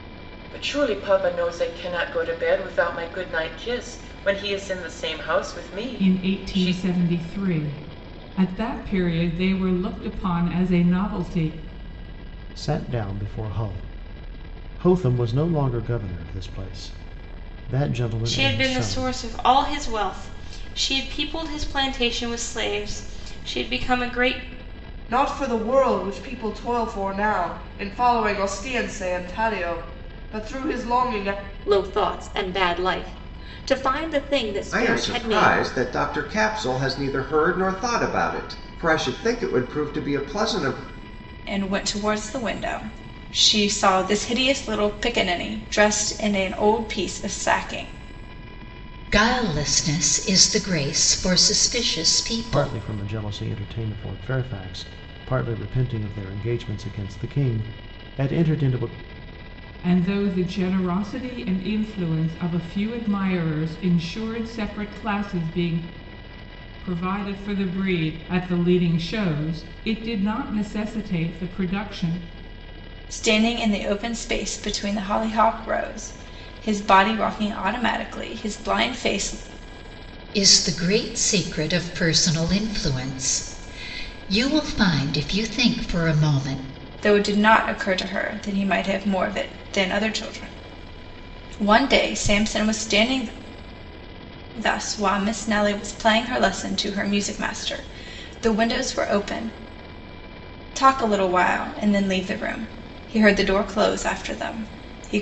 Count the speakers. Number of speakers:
nine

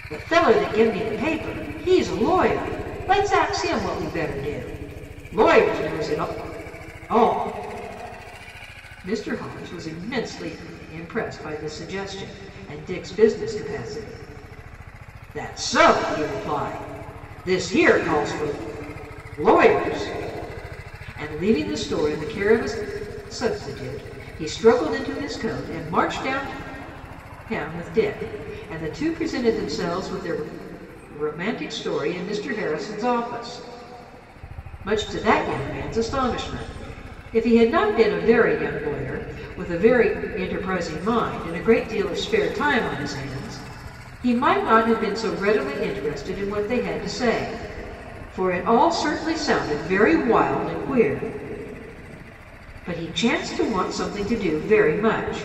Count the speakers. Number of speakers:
one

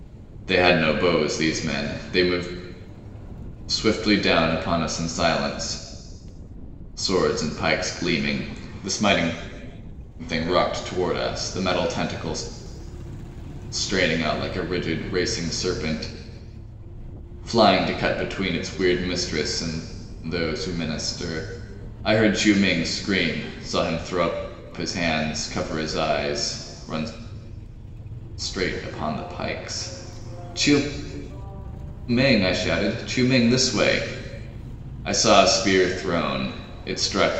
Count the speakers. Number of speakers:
one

